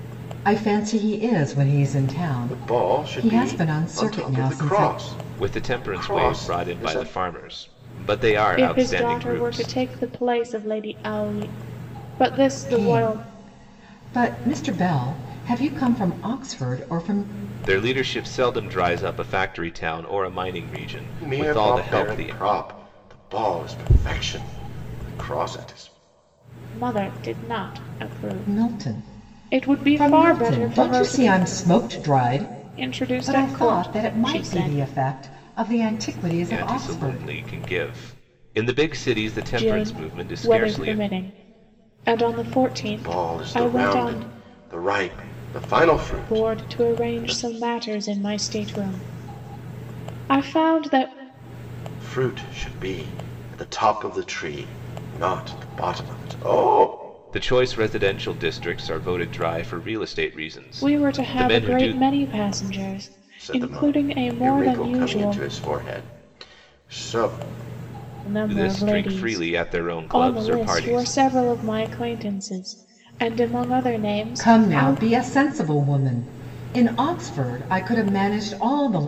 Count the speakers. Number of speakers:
4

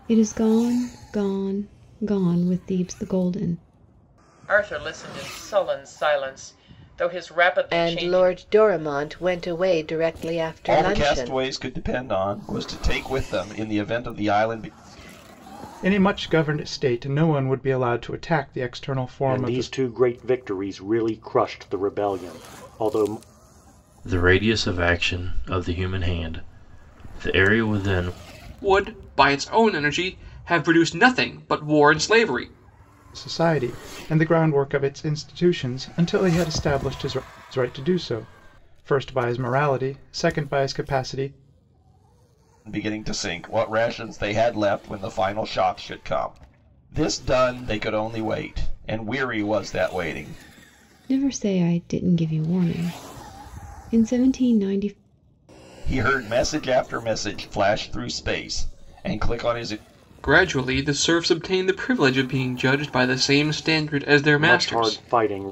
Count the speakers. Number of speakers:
8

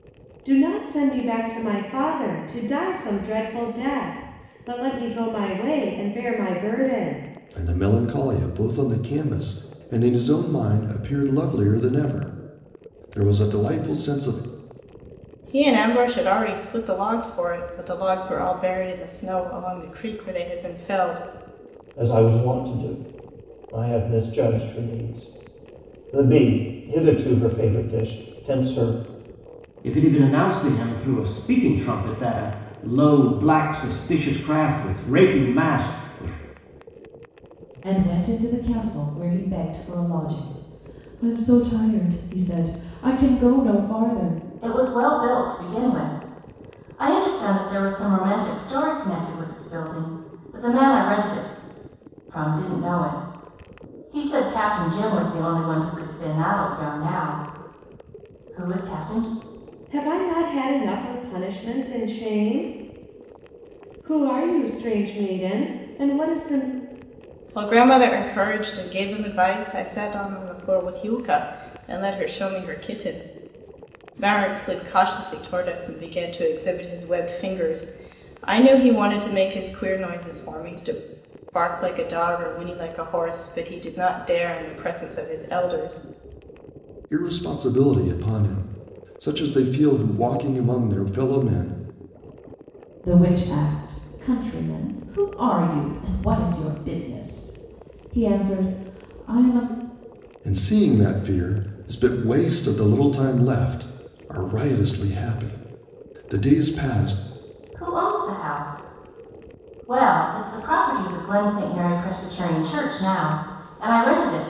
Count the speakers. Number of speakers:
7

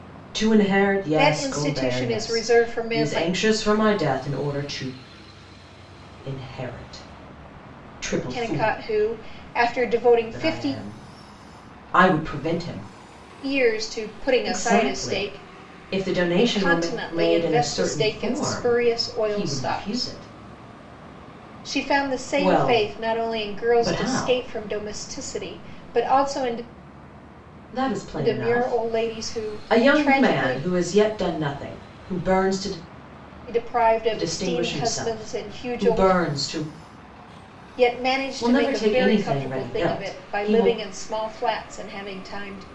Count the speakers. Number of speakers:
2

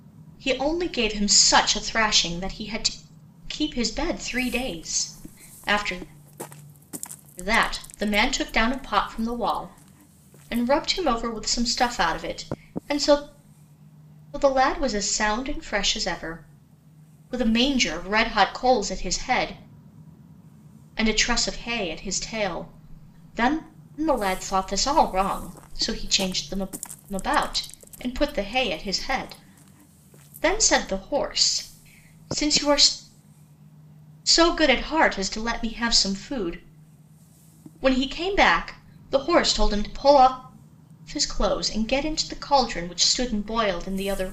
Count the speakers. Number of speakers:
1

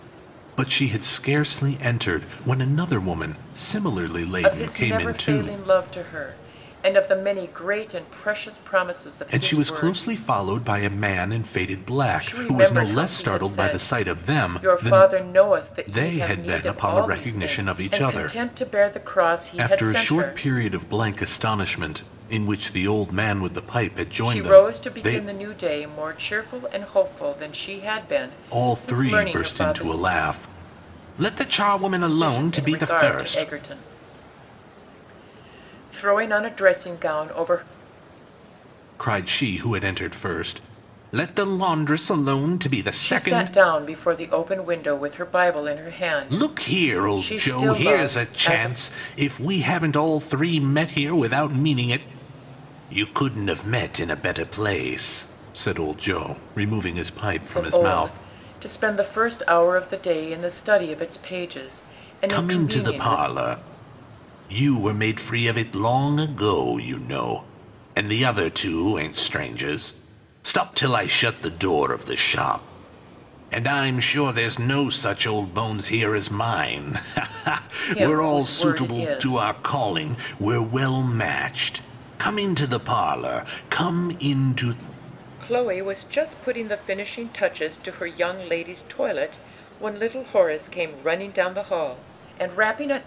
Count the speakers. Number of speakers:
2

